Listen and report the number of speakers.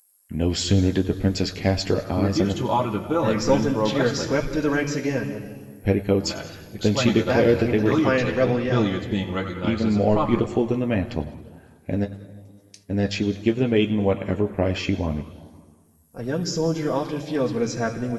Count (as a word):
three